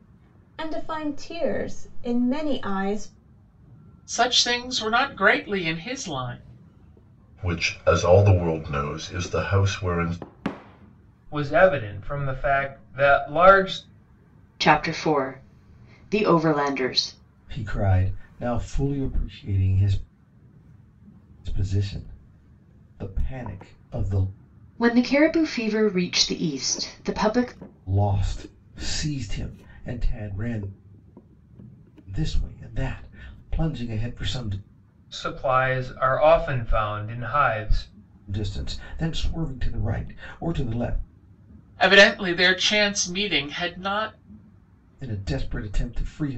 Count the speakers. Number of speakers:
six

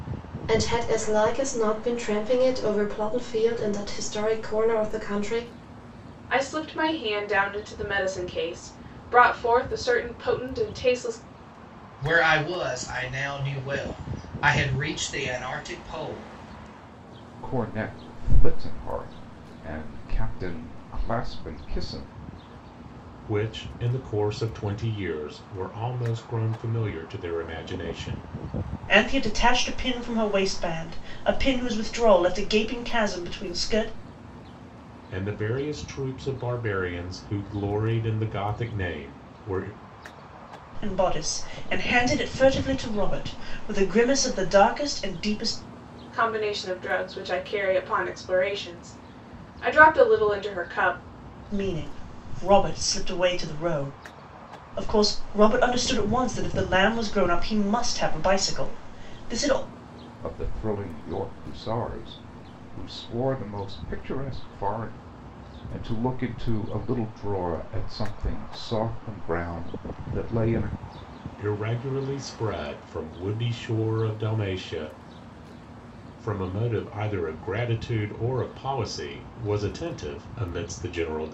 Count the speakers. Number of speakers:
six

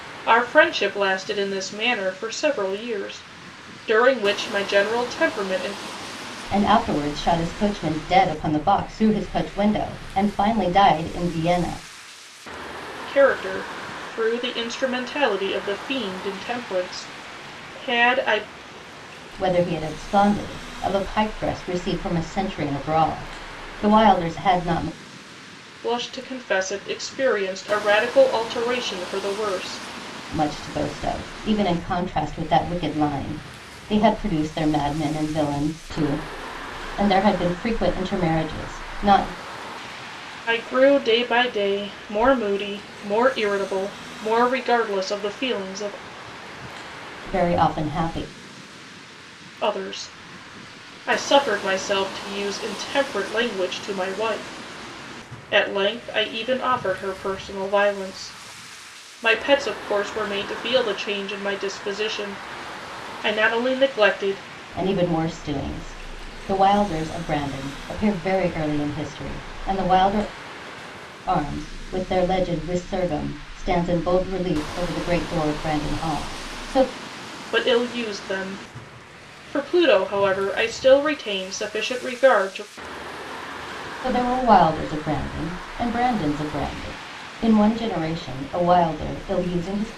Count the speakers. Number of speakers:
two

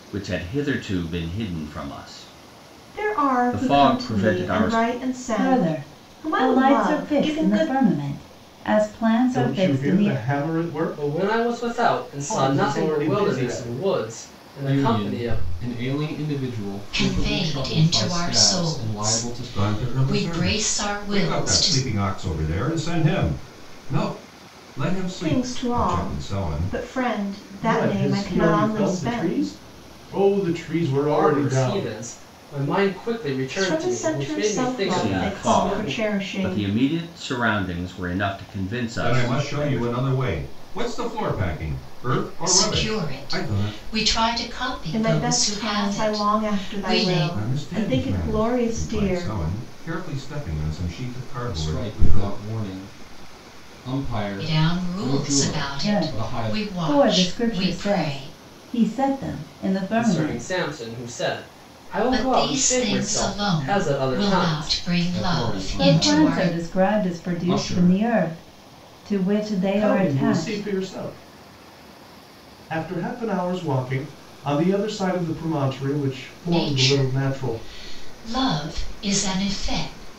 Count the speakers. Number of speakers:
eight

